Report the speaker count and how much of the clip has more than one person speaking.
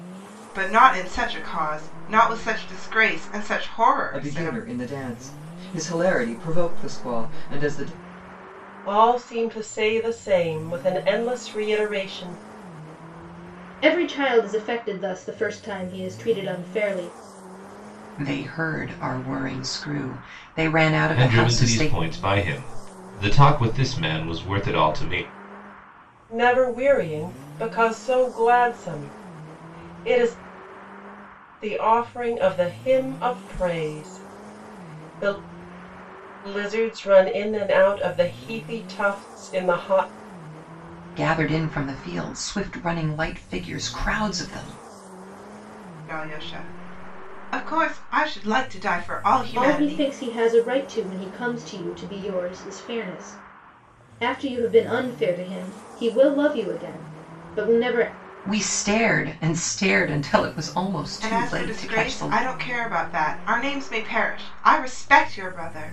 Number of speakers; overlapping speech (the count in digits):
6, about 5%